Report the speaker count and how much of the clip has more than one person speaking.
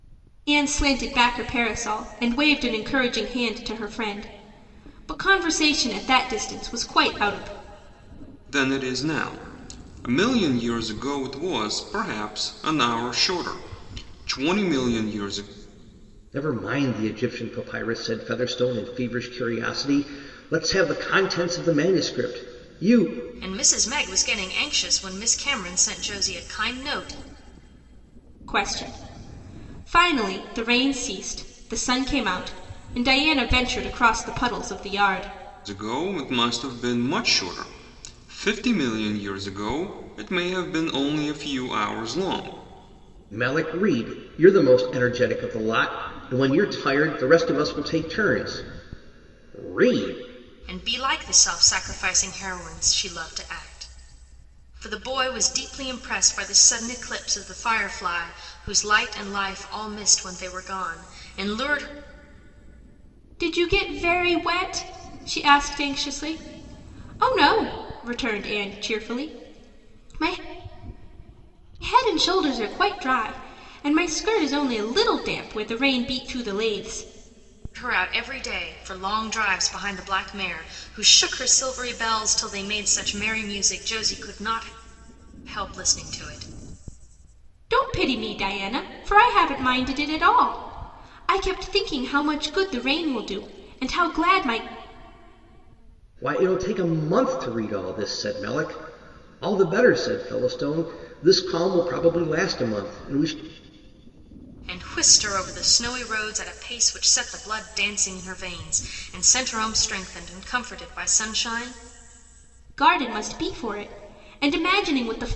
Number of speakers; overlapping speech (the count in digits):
4, no overlap